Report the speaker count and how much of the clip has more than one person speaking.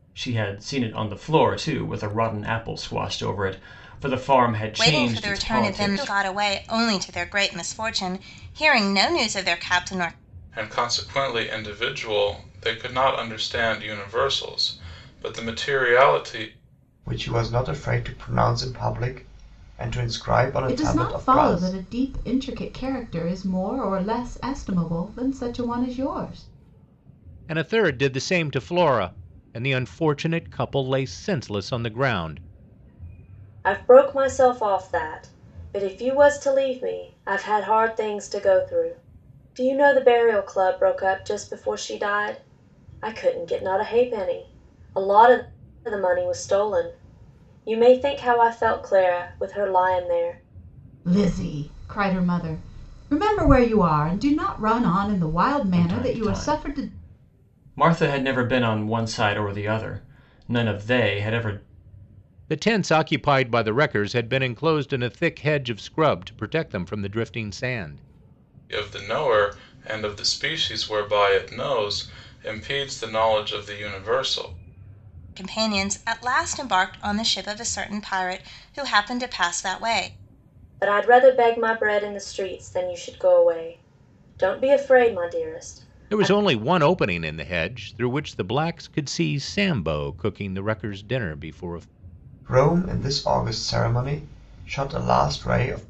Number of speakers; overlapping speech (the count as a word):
seven, about 4%